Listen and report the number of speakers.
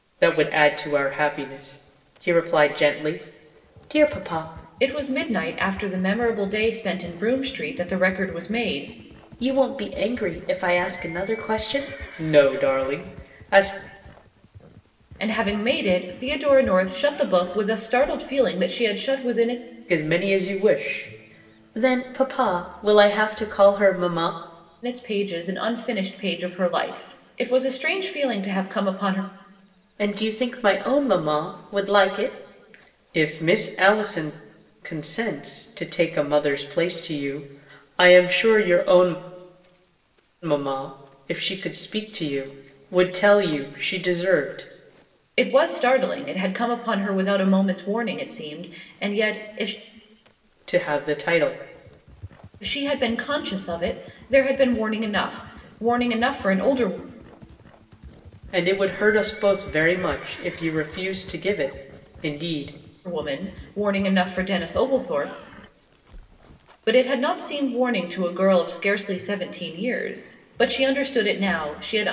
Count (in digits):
2